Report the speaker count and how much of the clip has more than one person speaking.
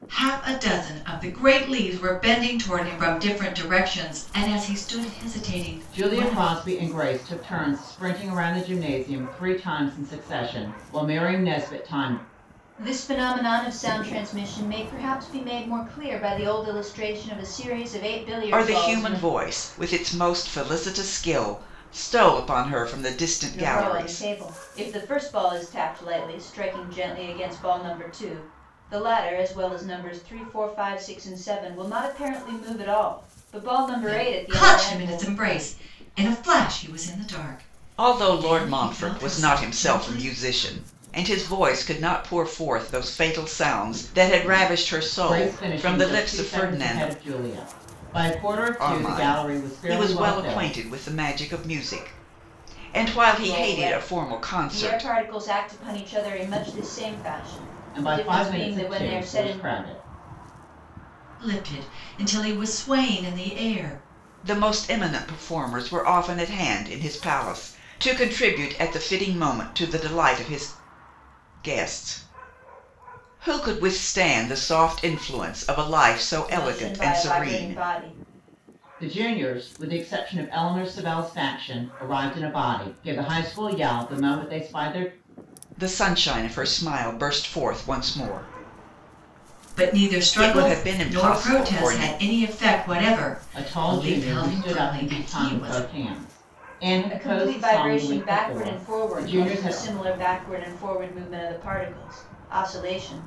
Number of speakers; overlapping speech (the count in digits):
4, about 22%